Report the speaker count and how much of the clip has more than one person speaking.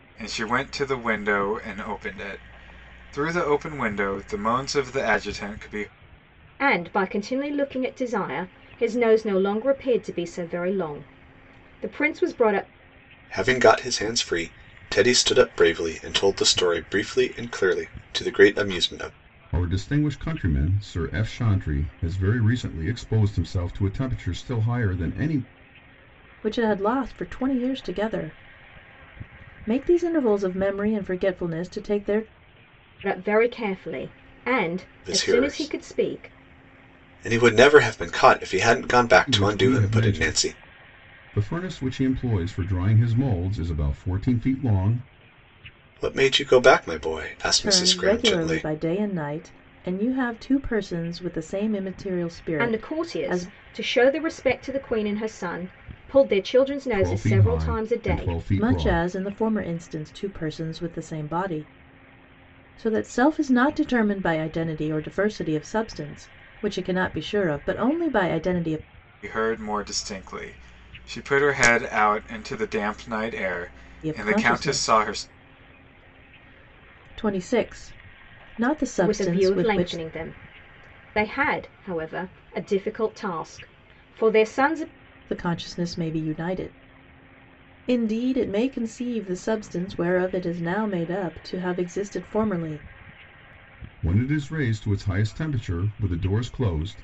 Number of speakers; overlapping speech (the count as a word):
five, about 9%